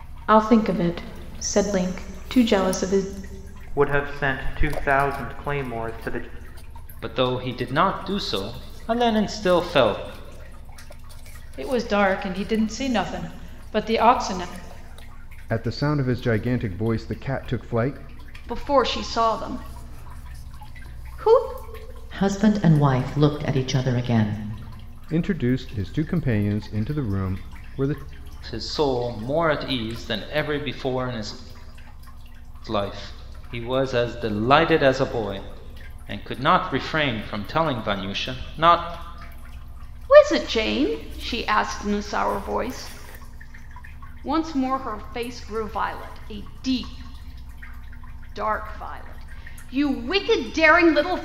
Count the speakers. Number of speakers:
seven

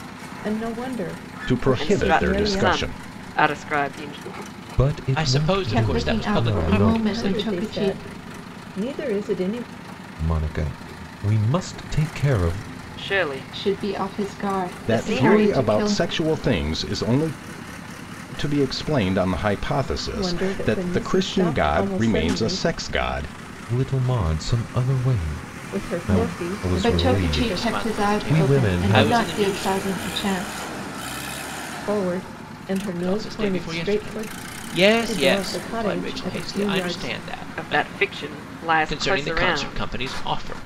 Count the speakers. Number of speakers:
six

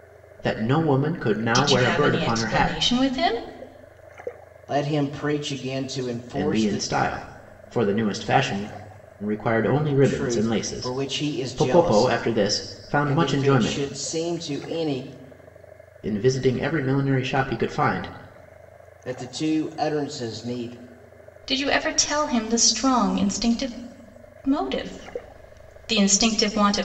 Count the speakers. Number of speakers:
three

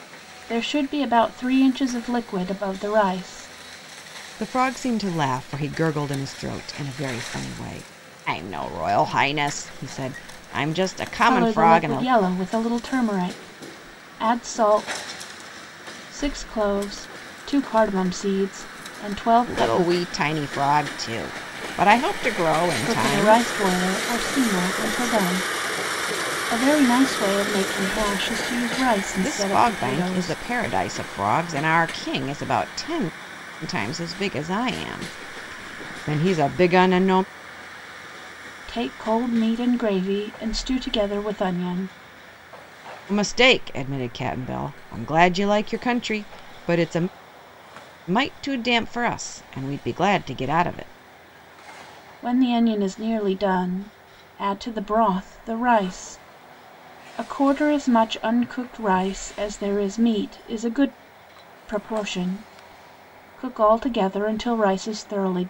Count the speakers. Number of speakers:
two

